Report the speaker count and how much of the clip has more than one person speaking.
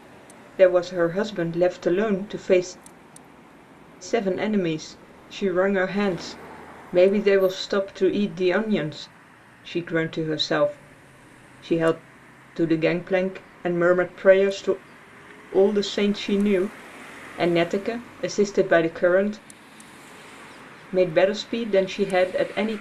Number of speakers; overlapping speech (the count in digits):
1, no overlap